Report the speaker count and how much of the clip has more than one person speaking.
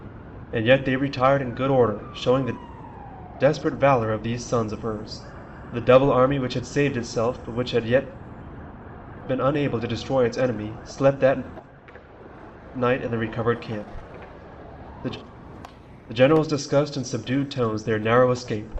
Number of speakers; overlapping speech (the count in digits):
1, no overlap